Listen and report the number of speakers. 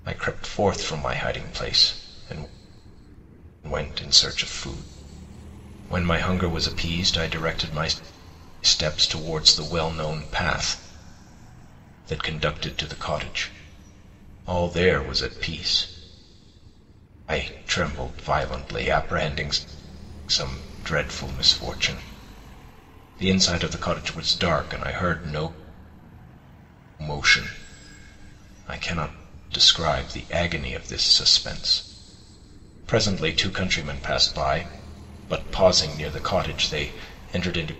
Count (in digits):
1